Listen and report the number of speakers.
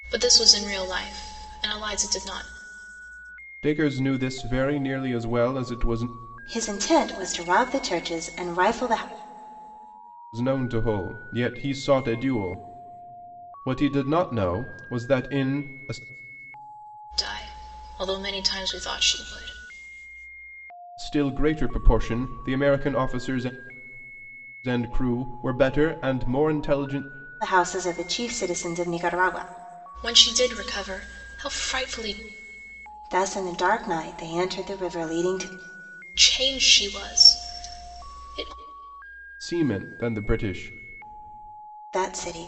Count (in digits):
3